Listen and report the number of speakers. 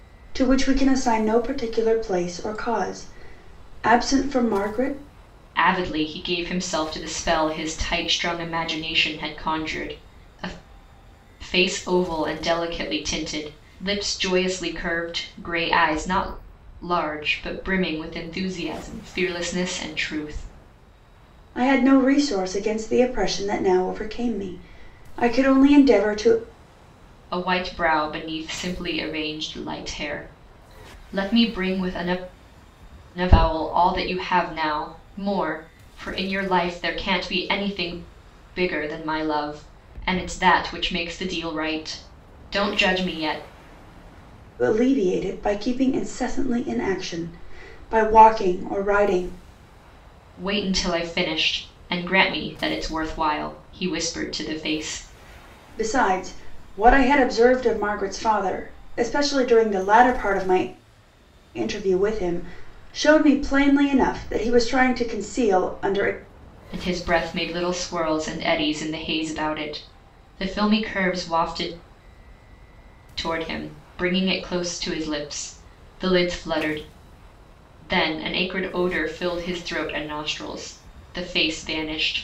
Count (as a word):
two